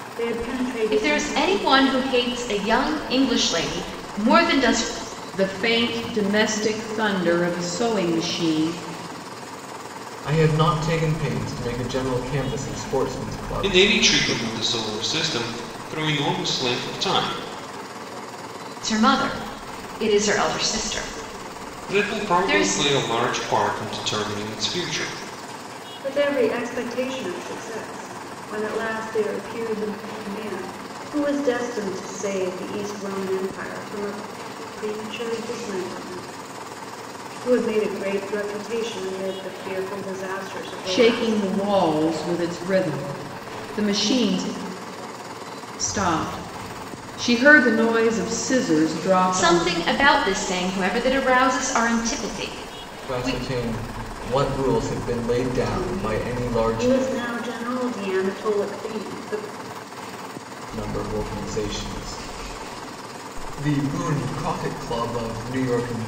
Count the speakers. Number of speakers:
5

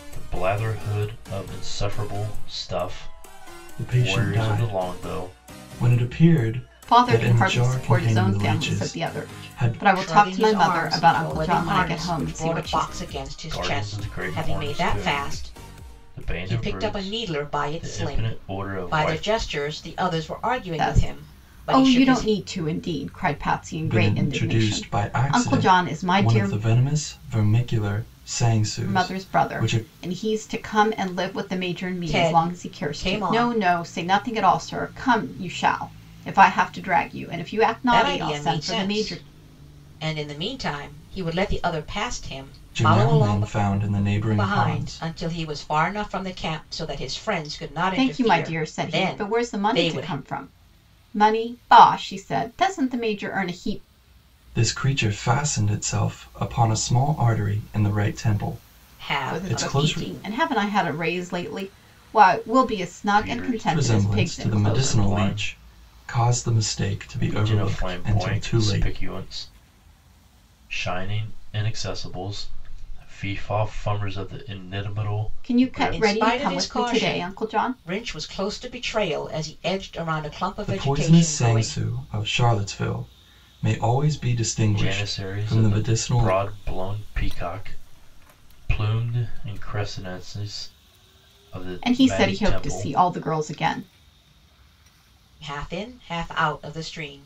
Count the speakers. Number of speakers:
4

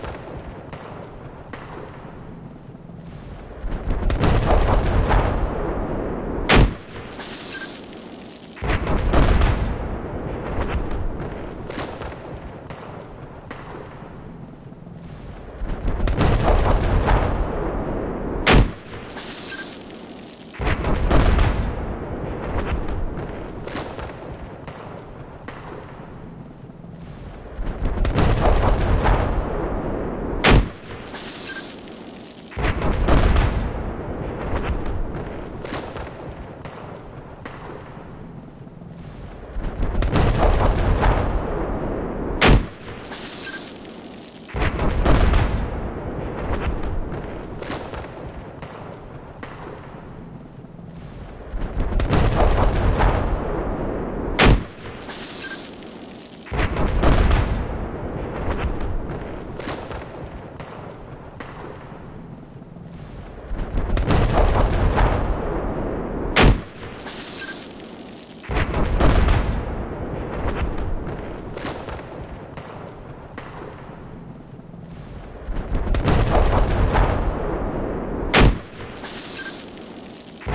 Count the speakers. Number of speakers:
0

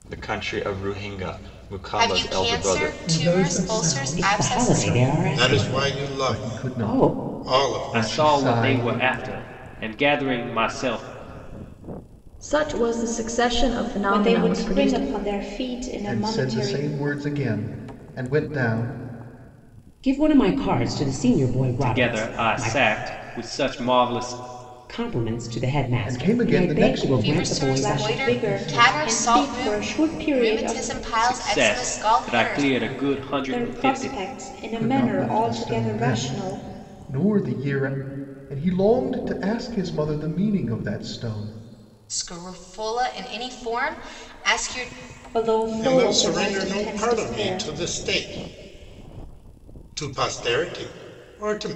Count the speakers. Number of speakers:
9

